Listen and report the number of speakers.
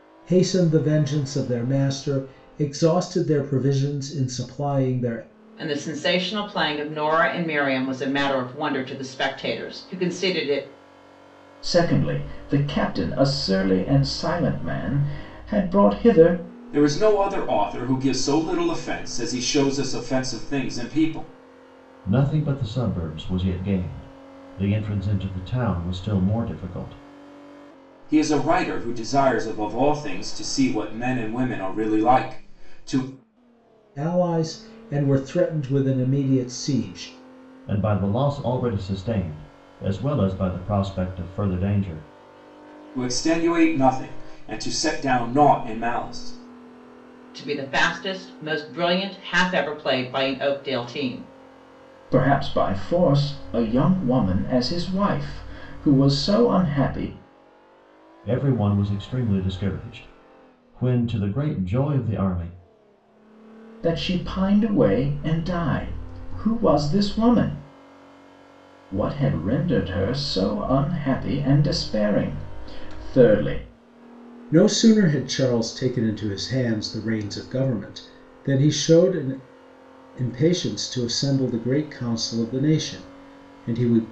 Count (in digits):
5